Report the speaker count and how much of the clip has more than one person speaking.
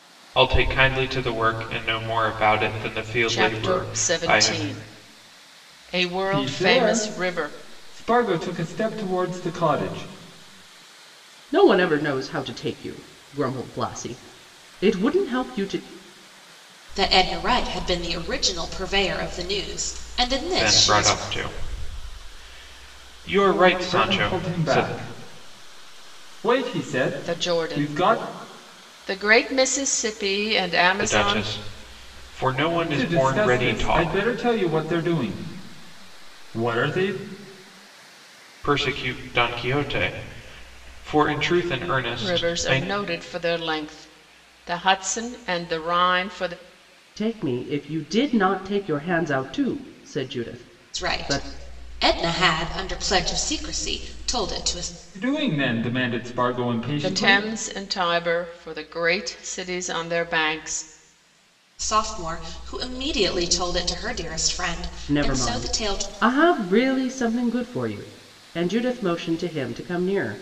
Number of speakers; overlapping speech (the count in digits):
5, about 15%